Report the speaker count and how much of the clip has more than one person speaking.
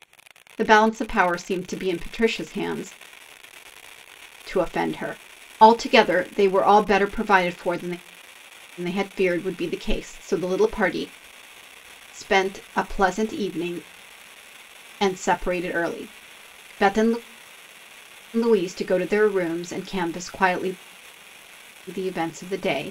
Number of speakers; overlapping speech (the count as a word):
one, no overlap